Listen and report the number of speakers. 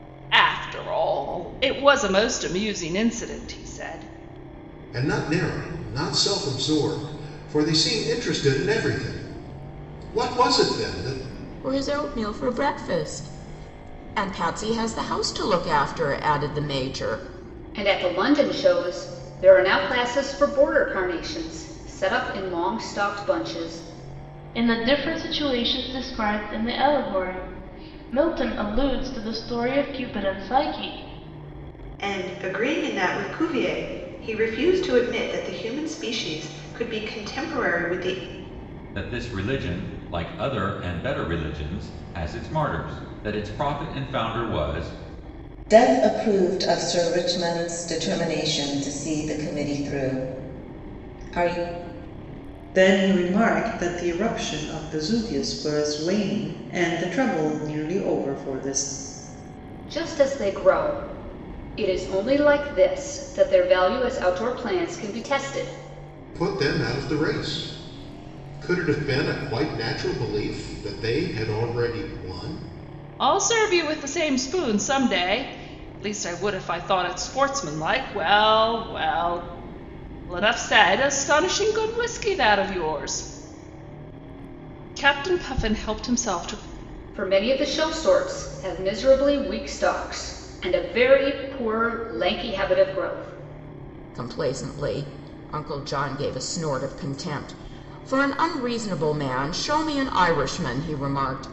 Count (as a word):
nine